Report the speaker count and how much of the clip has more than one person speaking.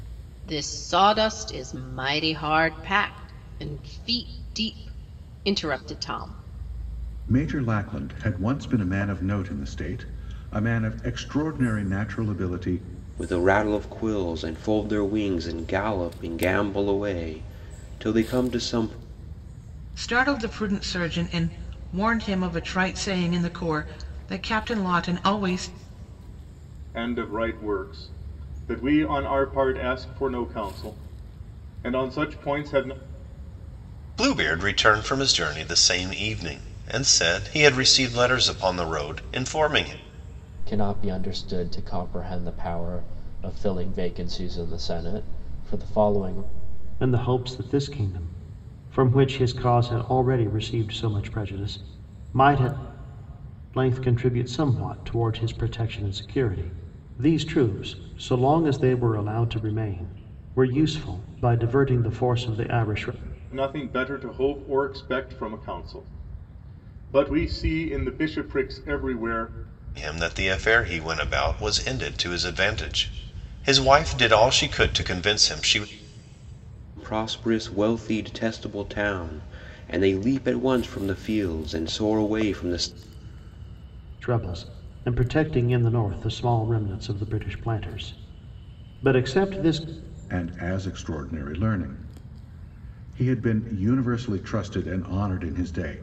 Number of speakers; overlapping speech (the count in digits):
8, no overlap